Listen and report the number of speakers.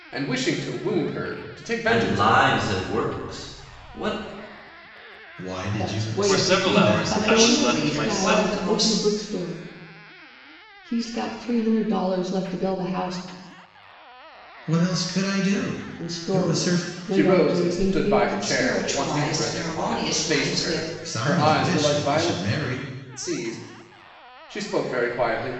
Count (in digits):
6